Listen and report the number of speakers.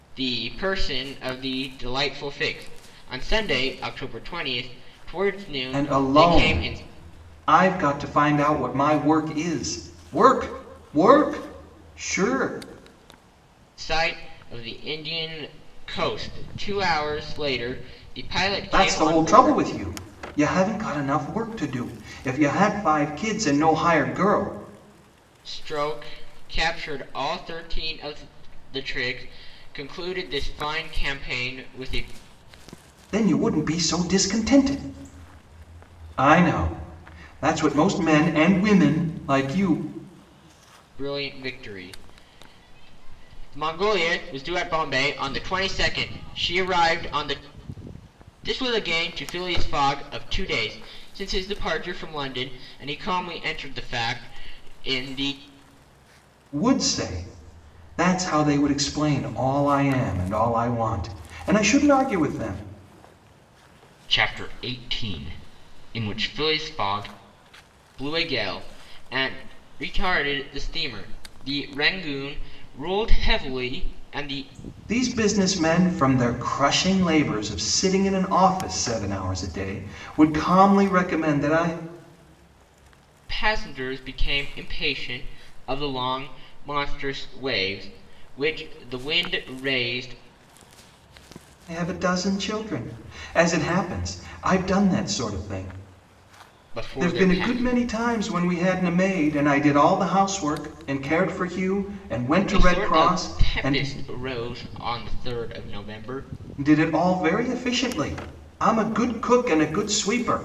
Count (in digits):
2